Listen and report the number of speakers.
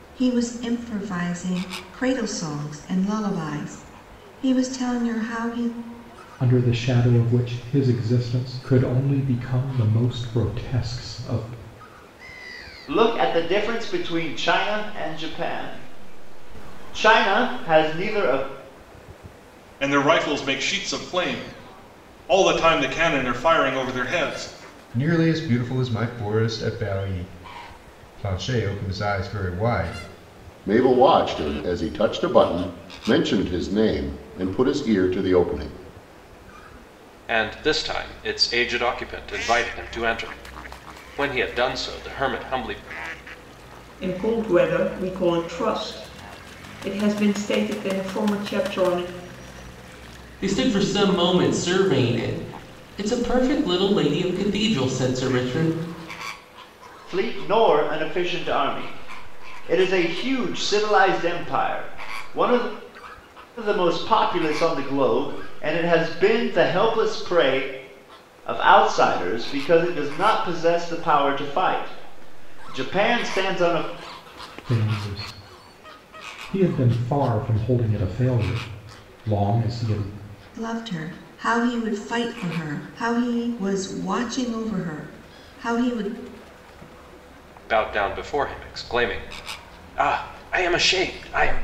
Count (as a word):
nine